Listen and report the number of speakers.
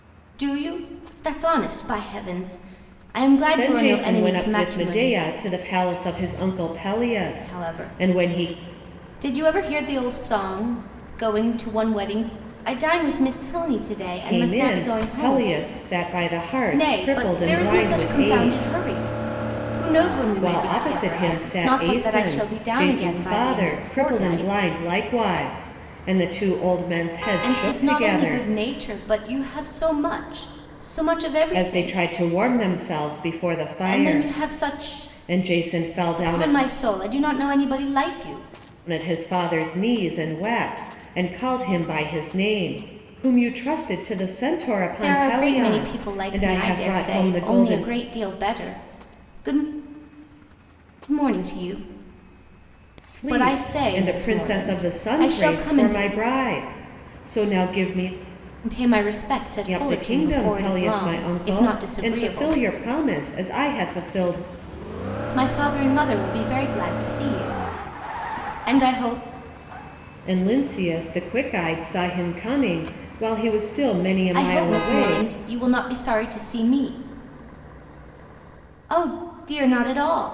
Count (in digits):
2